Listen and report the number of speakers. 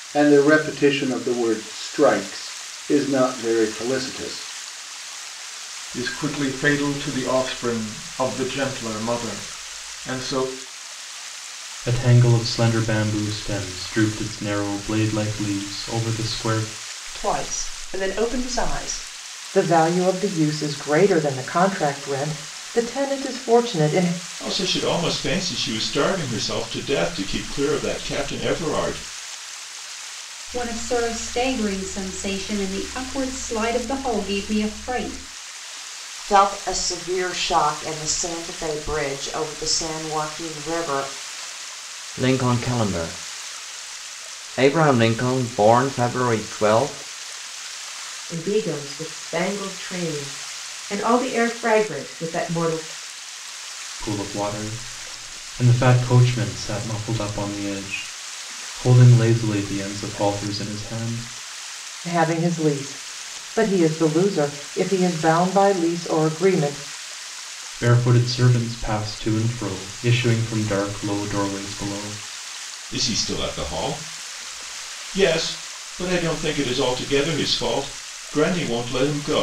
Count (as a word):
ten